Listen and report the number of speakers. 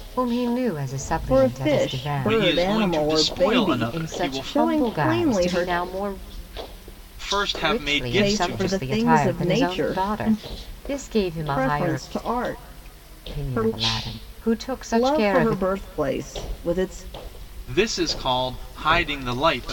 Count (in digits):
3